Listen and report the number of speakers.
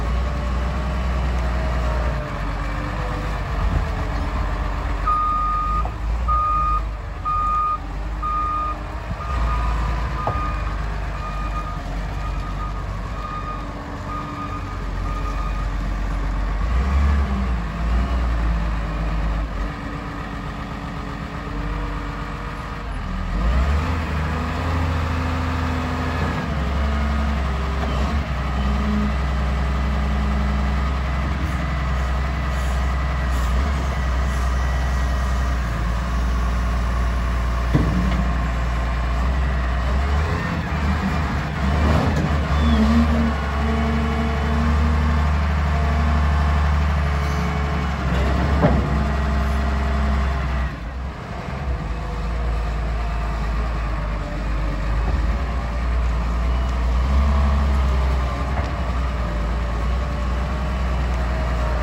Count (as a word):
zero